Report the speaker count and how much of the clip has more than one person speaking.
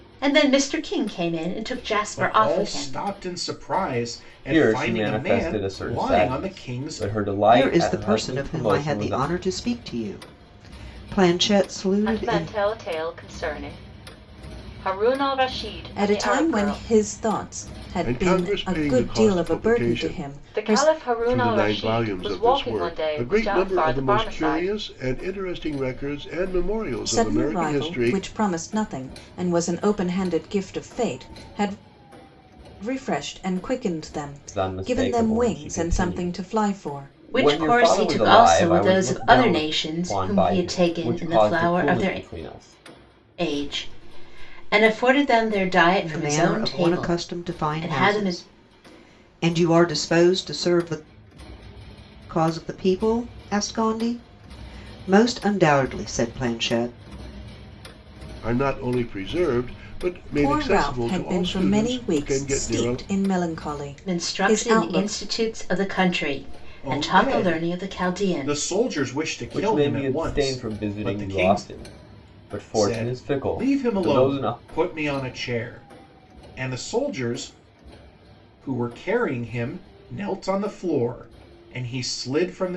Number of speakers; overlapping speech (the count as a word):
seven, about 41%